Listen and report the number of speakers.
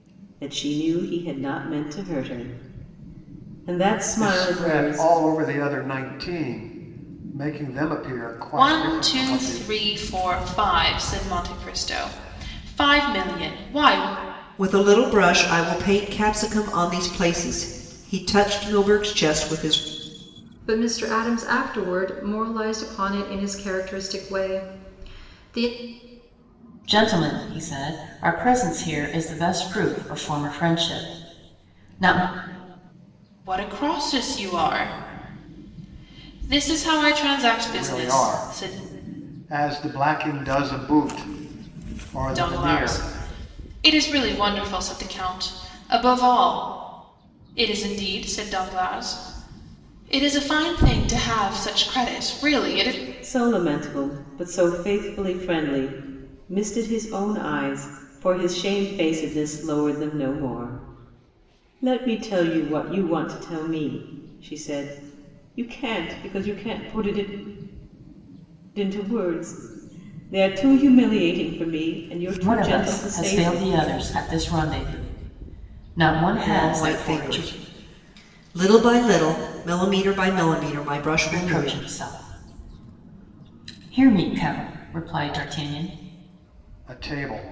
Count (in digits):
6